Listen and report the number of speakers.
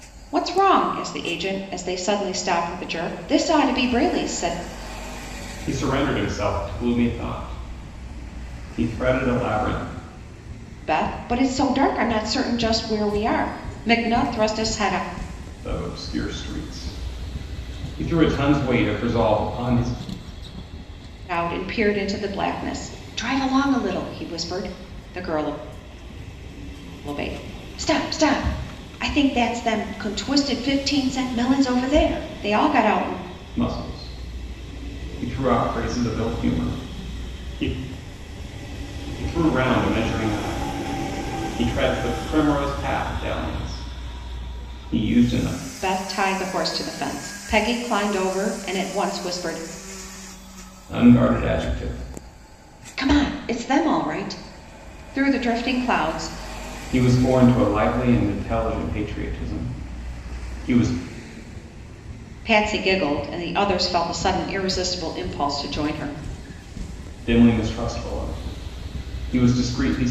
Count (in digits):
2